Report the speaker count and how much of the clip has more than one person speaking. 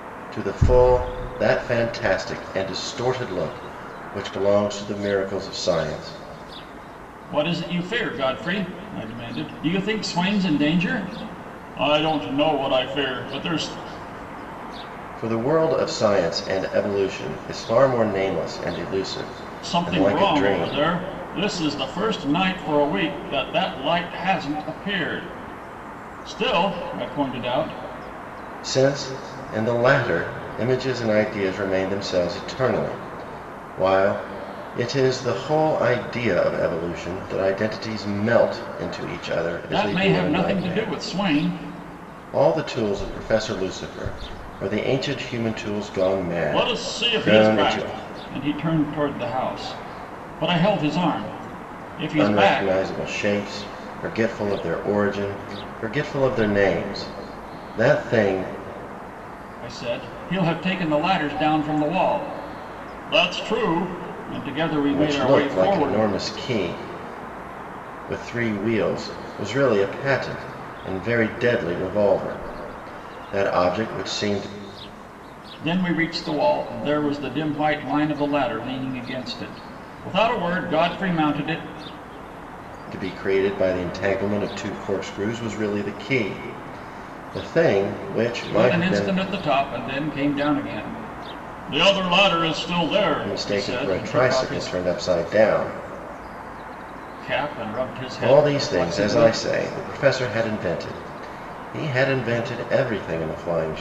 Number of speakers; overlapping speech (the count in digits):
2, about 9%